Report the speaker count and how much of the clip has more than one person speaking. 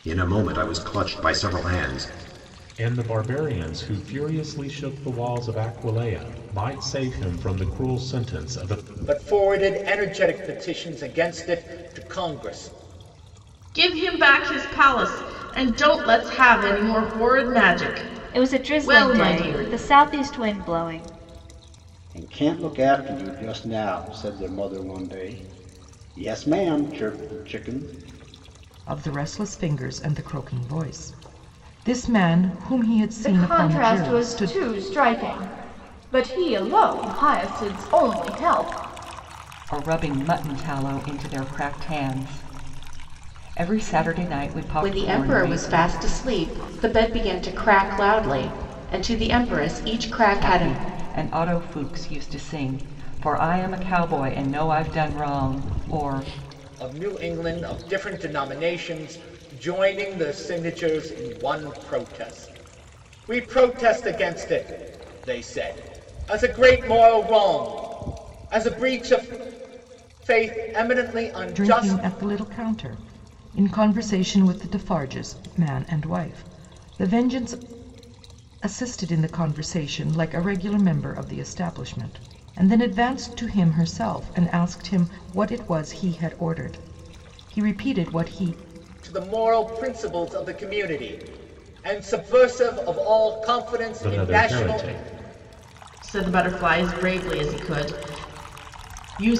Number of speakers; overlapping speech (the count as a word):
ten, about 6%